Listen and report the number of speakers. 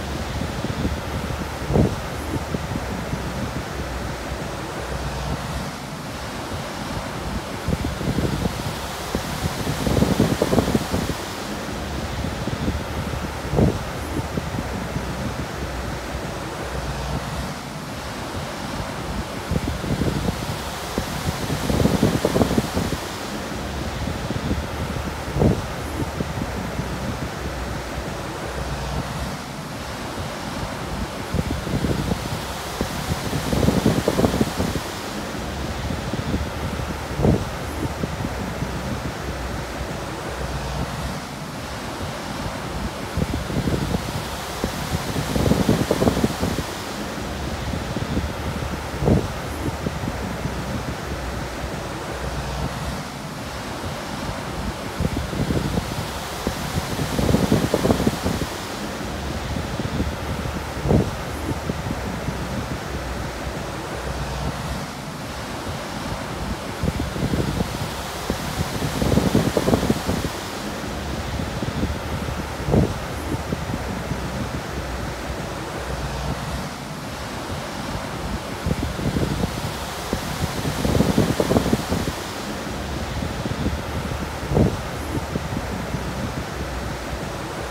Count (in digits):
0